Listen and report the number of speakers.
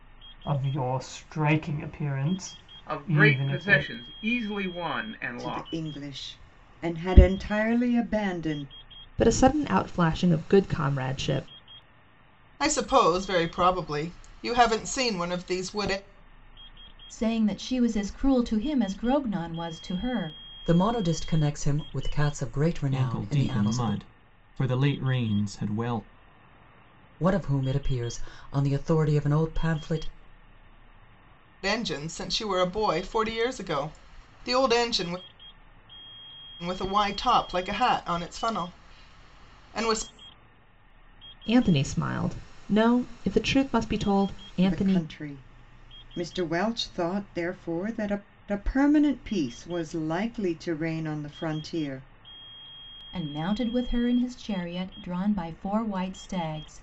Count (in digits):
8